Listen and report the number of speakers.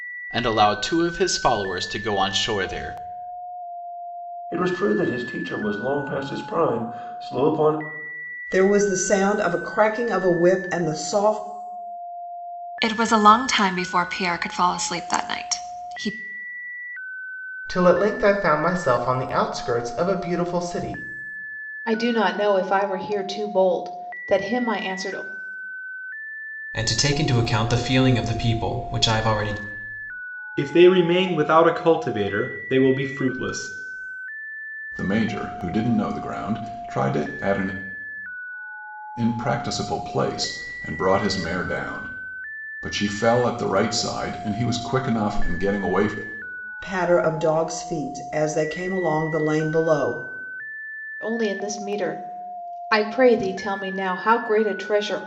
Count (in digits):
9